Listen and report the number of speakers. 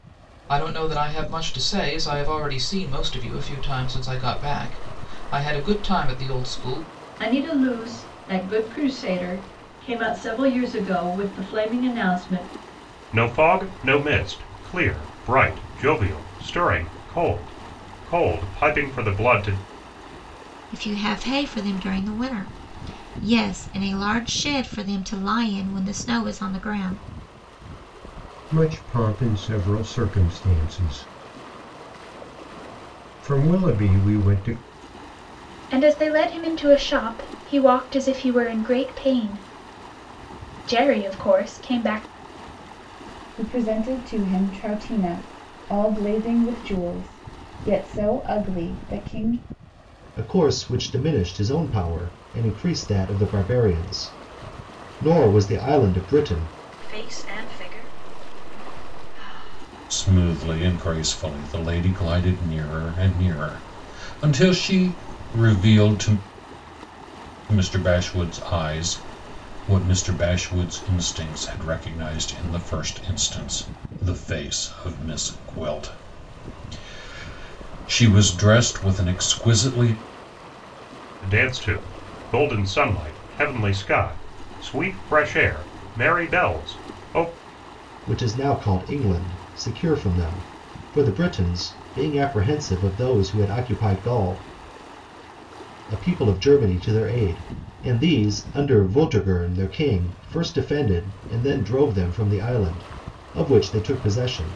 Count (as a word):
ten